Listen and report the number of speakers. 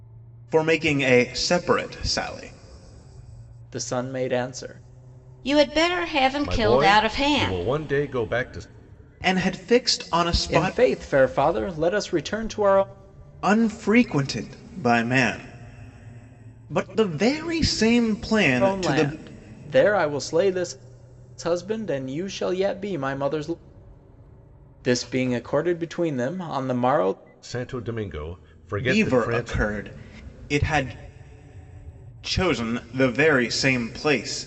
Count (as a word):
four